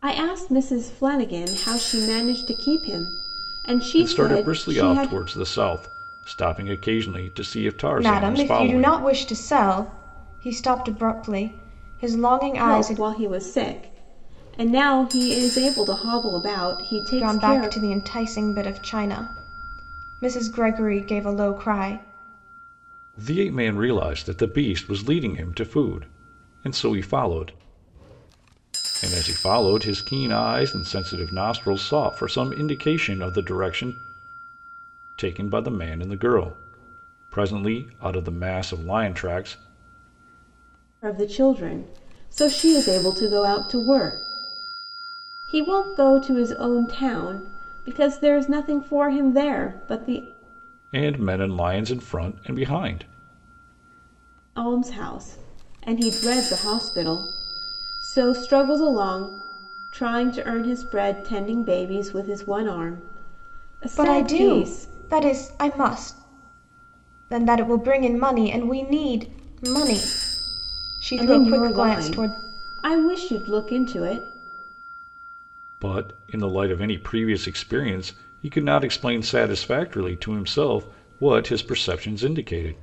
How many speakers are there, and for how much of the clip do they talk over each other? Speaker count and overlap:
3, about 7%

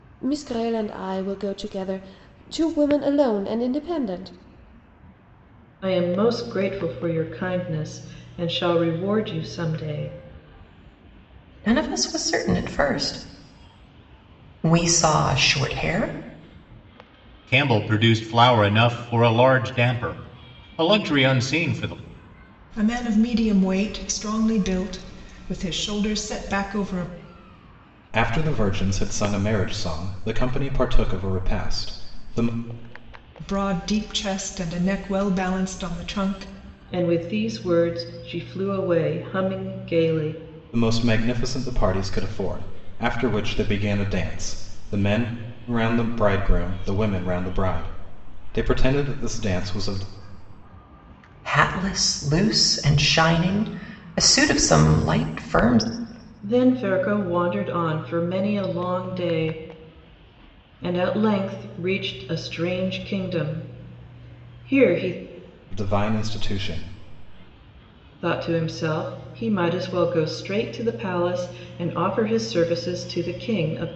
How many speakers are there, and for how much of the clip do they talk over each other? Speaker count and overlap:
6, no overlap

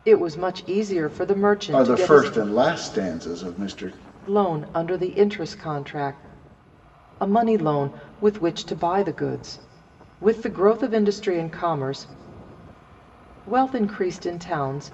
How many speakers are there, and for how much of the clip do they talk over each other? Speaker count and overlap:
2, about 4%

